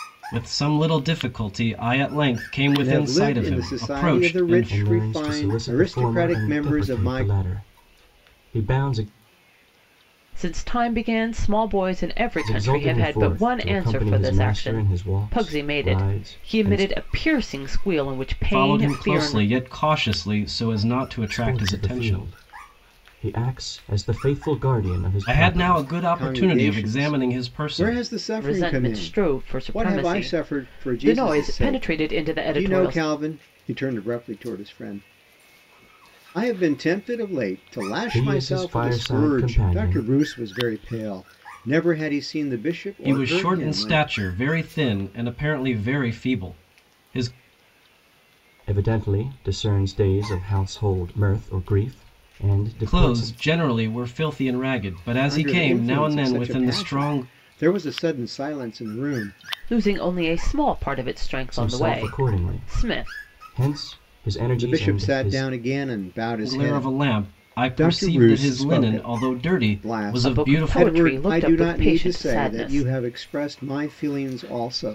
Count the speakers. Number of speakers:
4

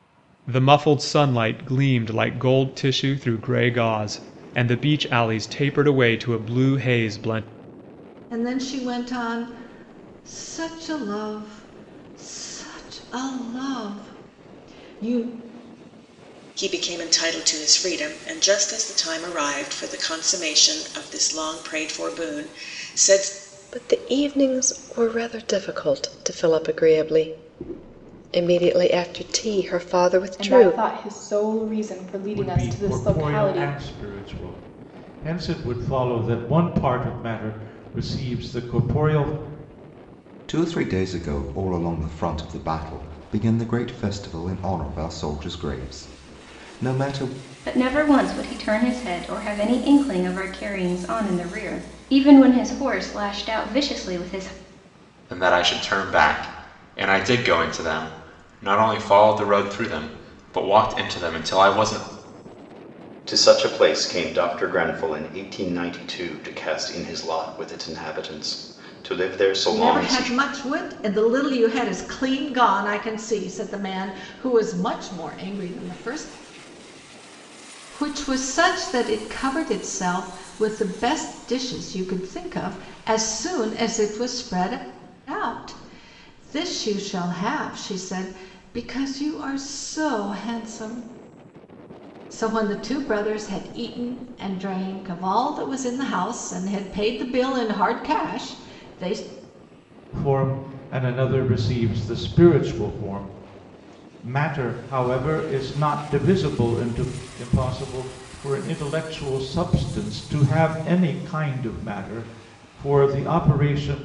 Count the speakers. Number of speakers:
10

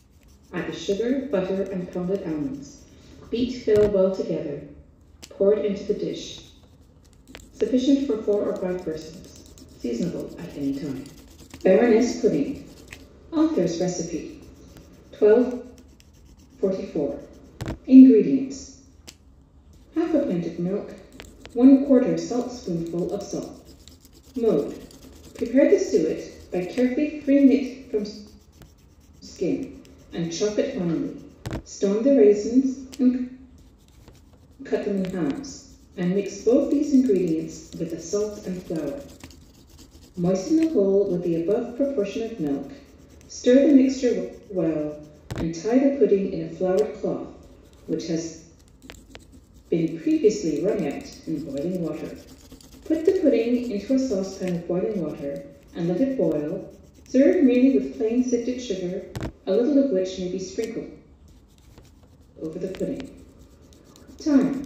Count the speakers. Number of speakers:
1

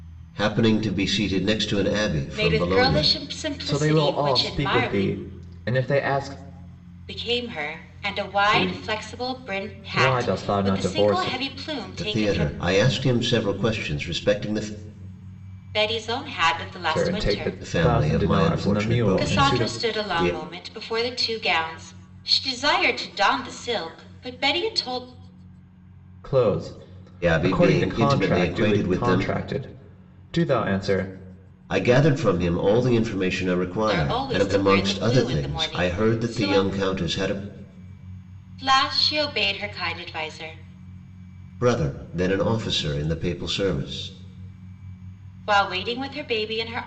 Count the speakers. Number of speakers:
3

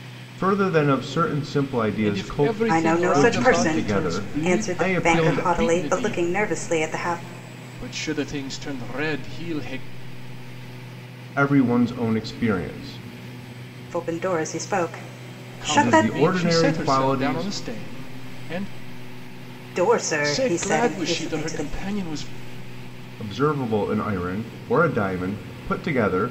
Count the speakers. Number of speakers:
3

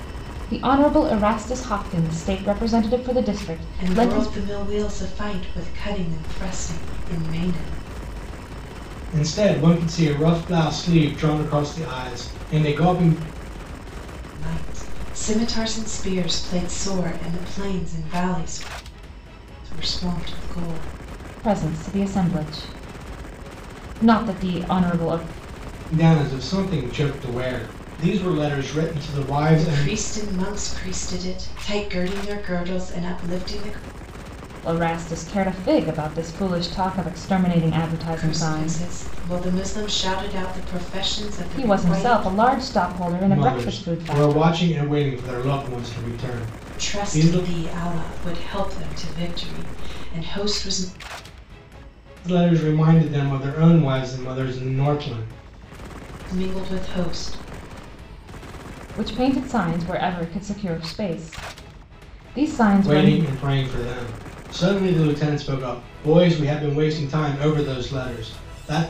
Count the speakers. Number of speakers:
3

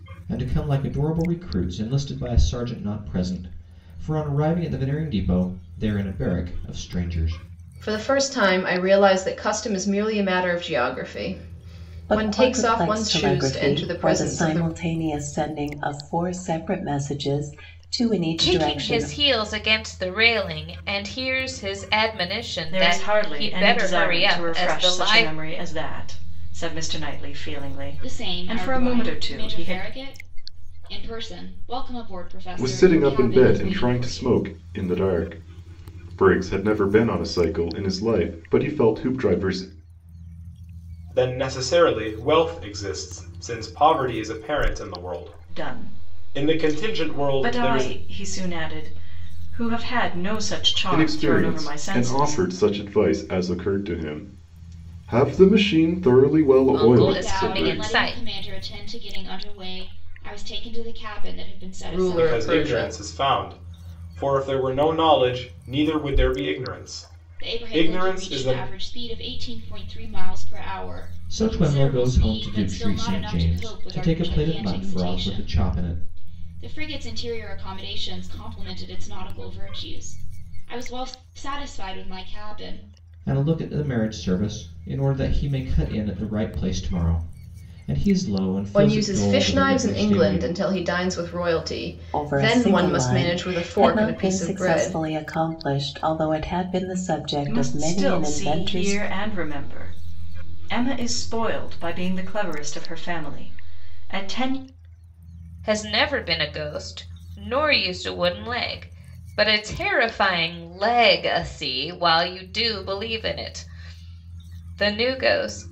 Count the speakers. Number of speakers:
8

